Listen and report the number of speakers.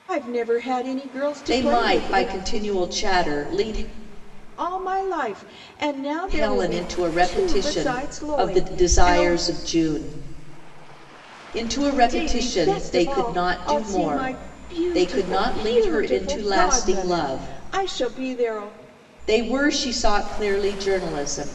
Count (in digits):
2